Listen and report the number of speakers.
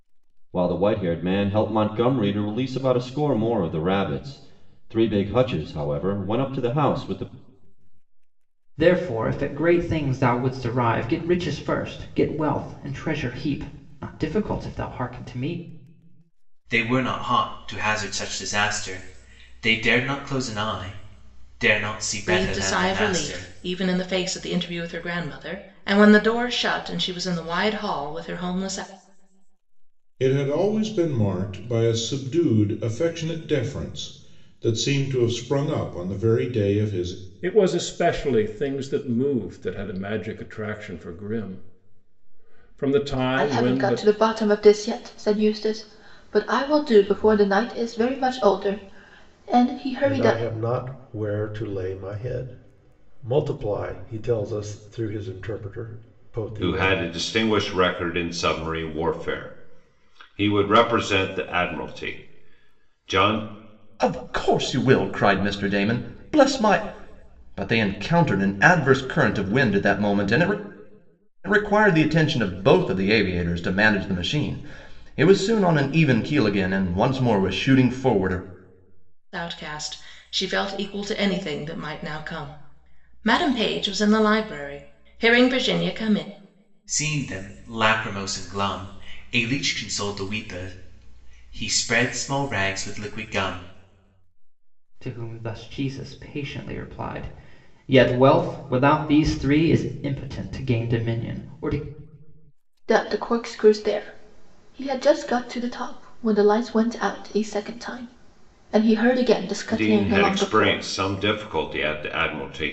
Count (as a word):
ten